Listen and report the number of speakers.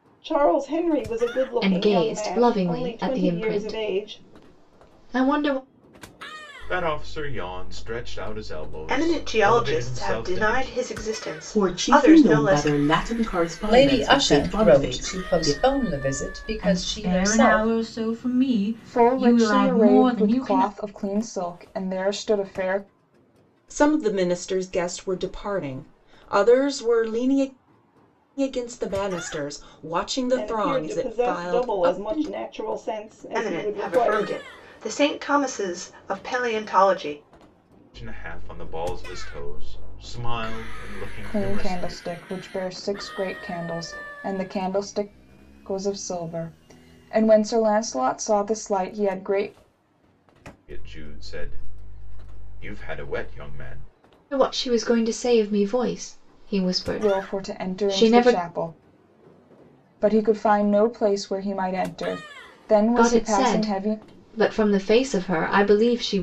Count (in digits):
9